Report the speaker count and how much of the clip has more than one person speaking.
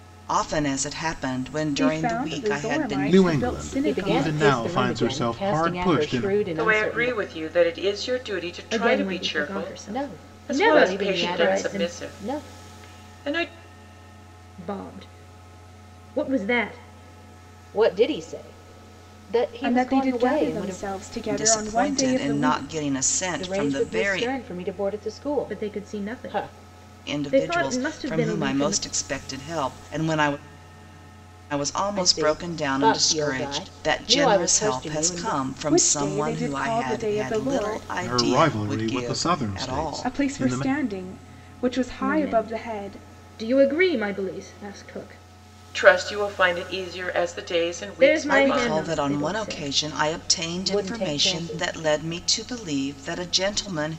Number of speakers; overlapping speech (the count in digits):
6, about 51%